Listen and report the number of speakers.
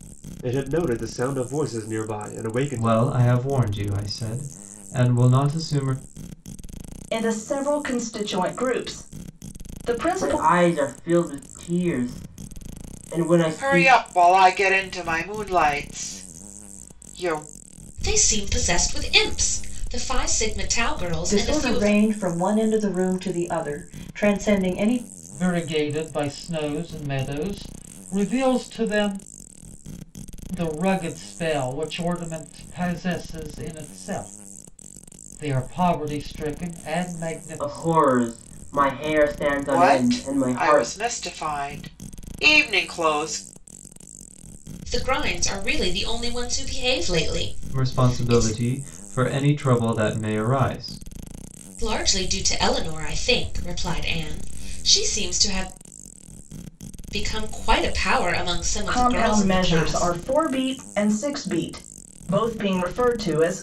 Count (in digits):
8